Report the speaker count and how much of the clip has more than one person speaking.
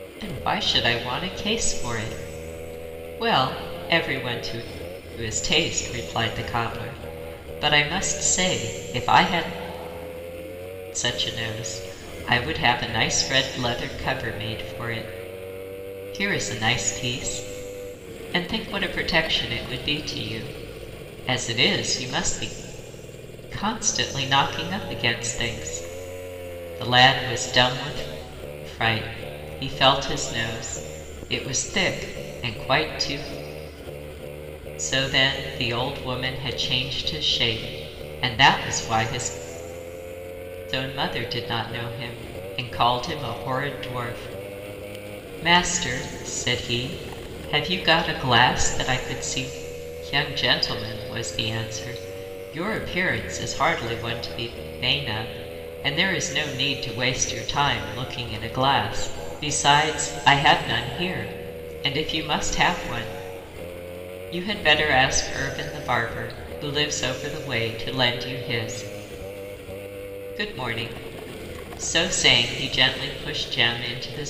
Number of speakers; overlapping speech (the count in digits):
1, no overlap